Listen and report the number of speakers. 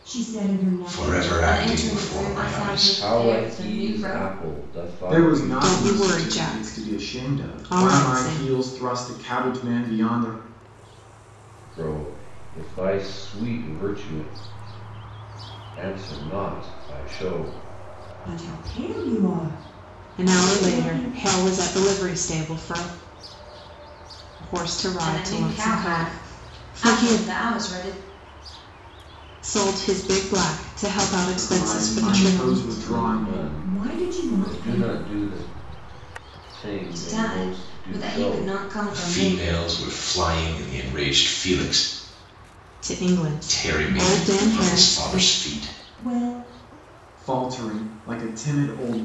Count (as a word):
six